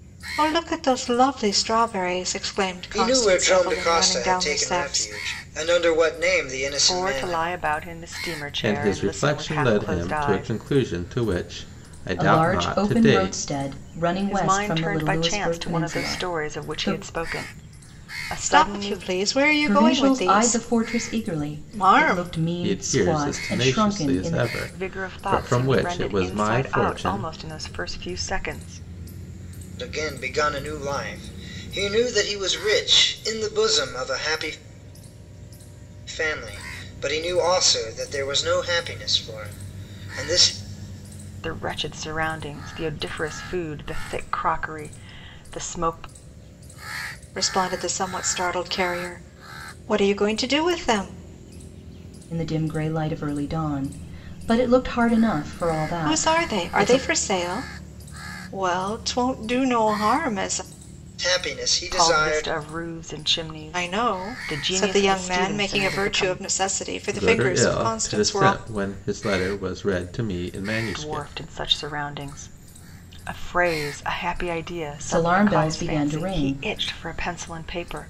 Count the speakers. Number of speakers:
5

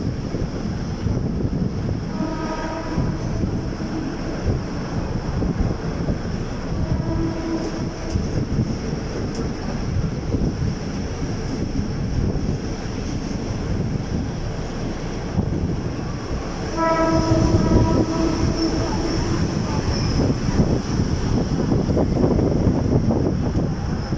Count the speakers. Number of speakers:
0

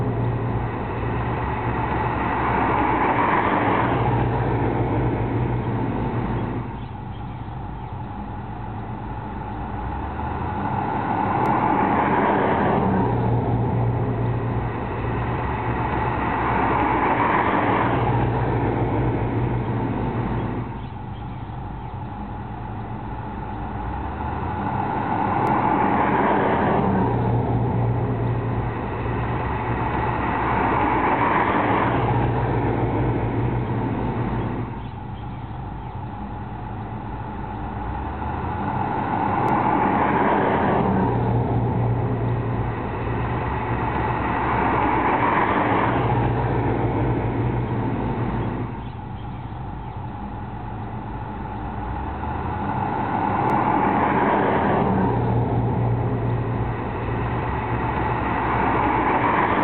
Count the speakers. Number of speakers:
0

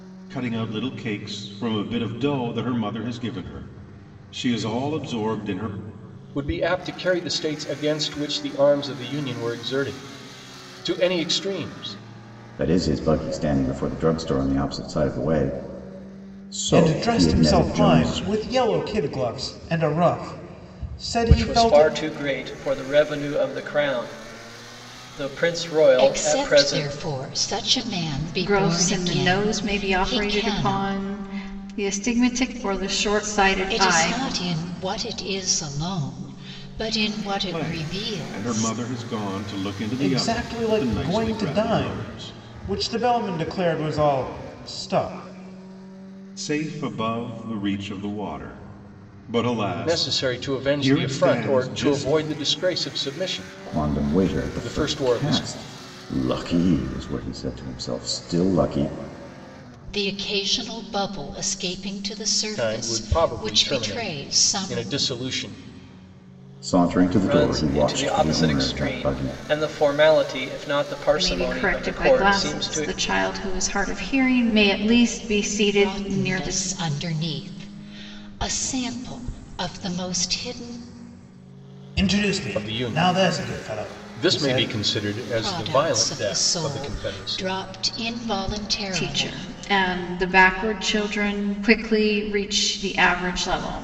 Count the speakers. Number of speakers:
7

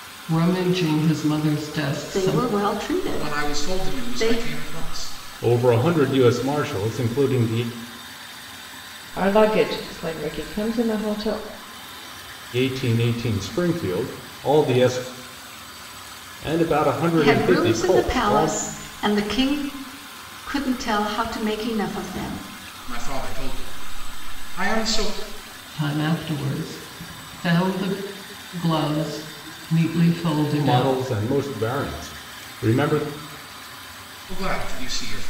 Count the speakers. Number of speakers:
5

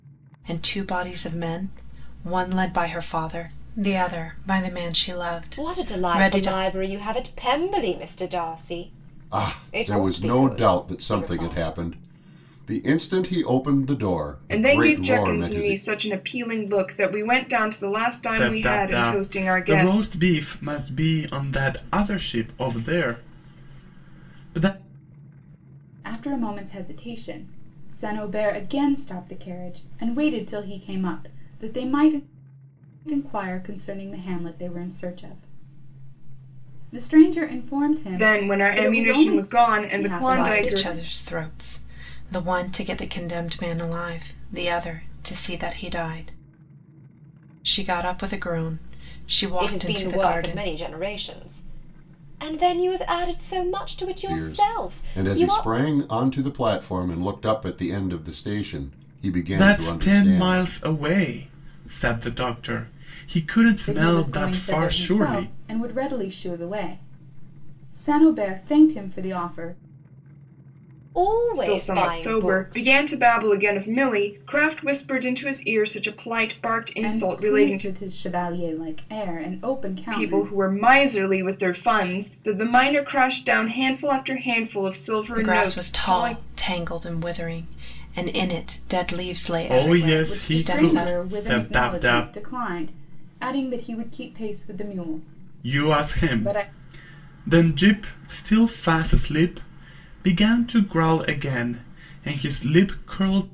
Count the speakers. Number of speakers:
6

